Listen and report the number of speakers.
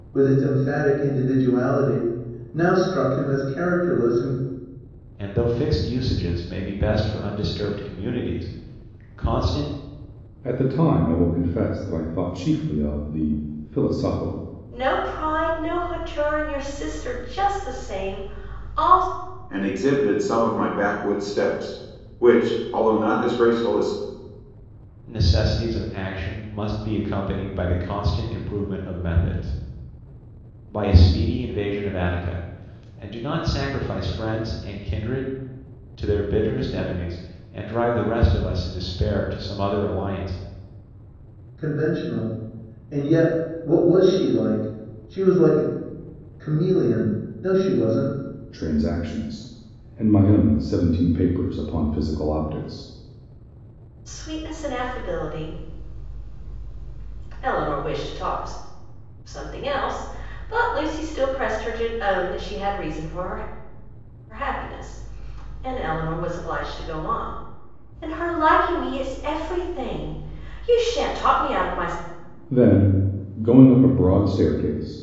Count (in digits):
5